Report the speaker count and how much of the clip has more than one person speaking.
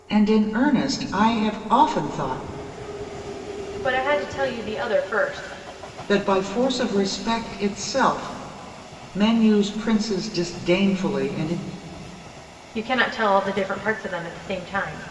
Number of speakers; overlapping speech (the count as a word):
two, no overlap